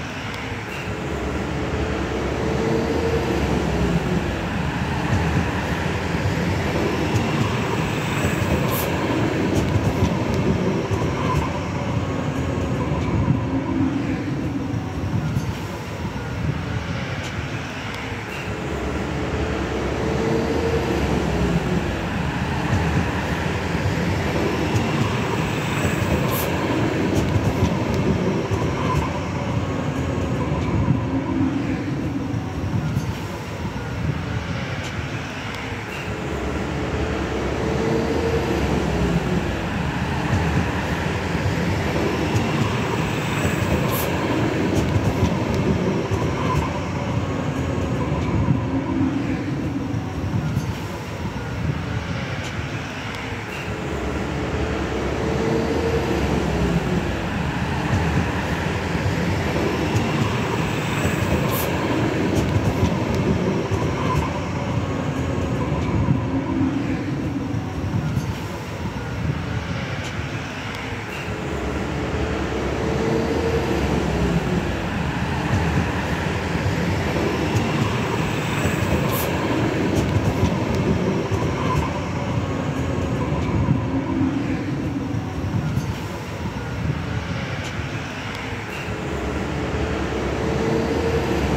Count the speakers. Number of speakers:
zero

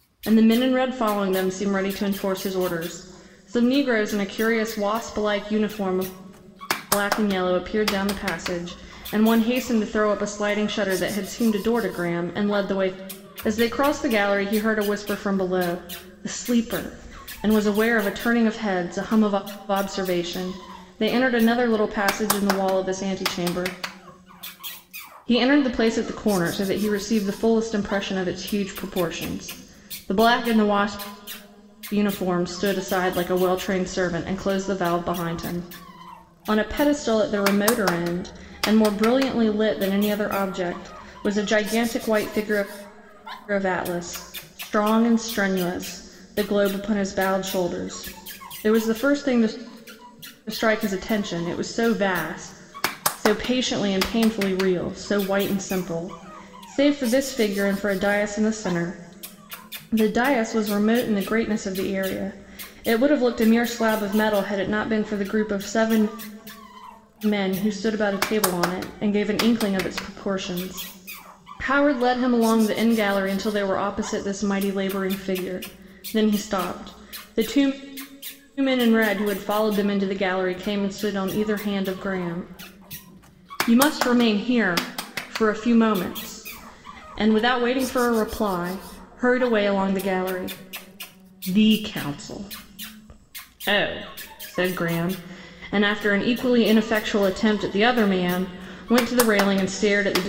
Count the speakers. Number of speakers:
one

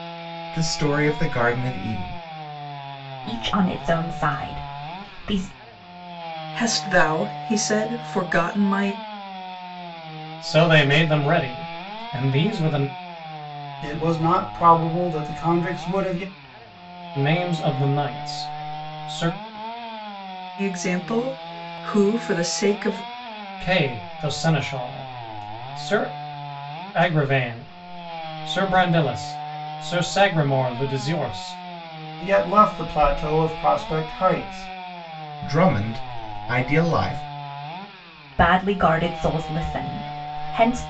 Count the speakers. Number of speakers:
five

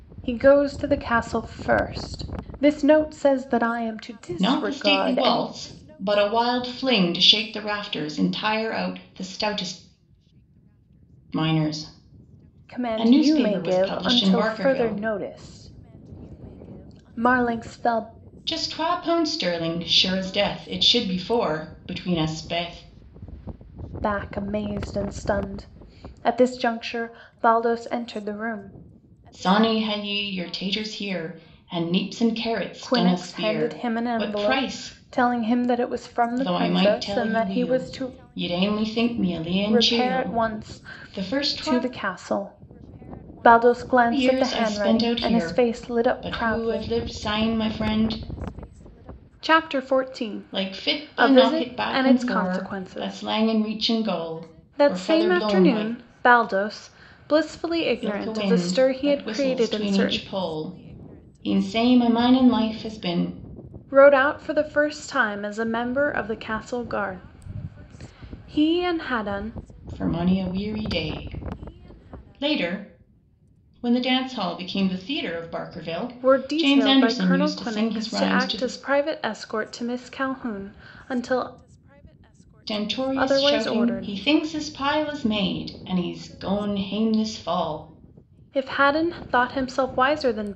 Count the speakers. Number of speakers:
two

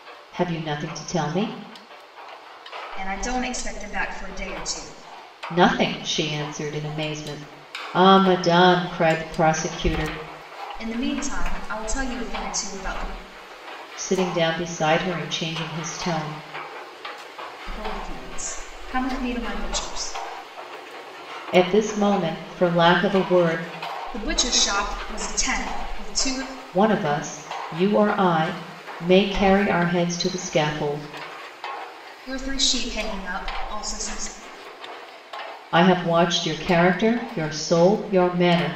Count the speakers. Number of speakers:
two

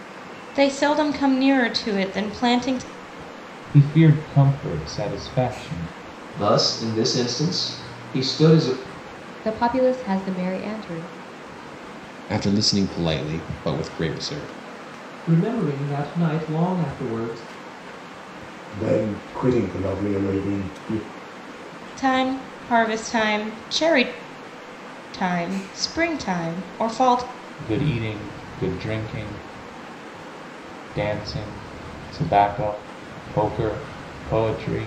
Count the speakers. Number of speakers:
seven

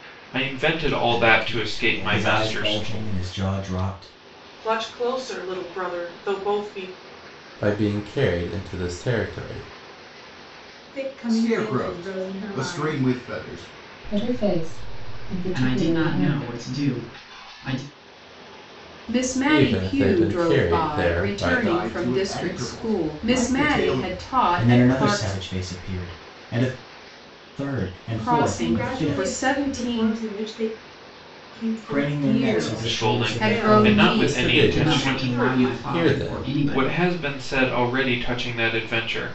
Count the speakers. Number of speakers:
ten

